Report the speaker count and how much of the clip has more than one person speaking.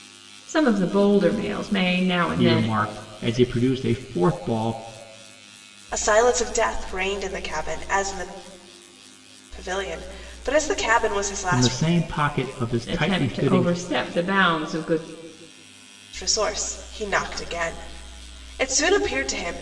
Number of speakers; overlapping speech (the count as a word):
three, about 9%